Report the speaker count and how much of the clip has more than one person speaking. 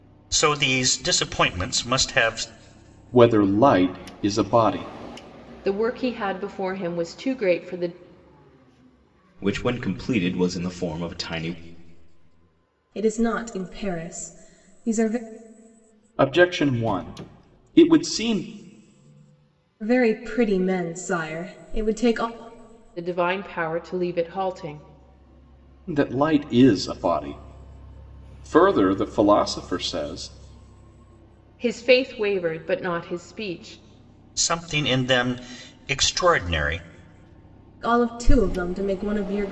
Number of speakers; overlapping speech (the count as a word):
five, no overlap